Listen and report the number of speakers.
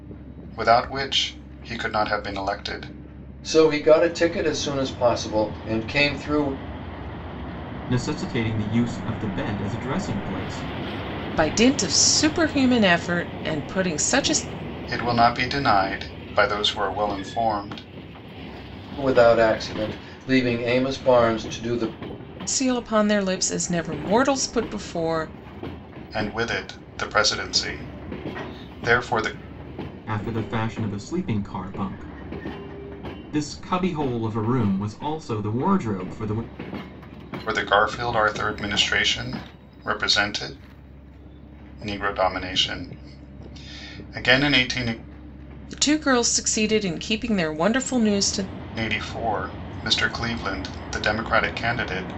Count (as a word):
four